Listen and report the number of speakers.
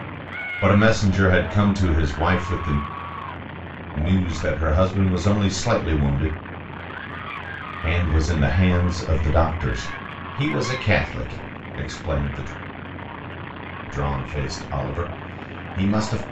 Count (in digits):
1